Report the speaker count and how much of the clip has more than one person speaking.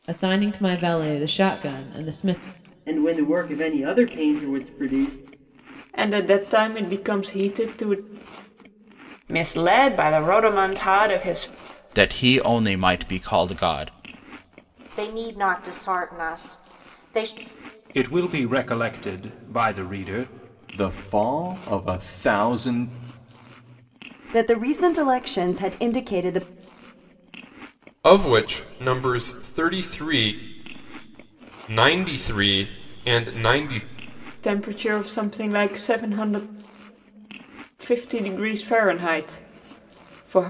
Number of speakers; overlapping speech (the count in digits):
10, no overlap